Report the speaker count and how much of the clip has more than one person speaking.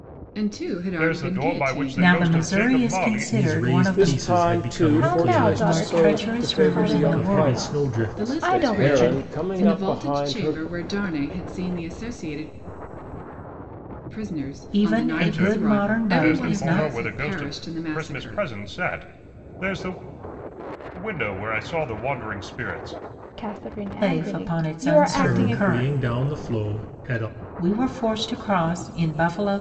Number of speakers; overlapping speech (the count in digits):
6, about 52%